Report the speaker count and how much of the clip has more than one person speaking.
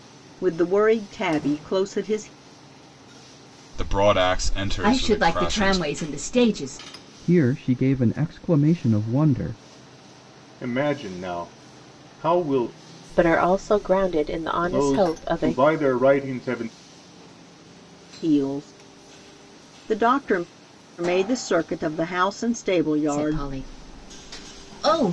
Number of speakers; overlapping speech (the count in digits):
6, about 9%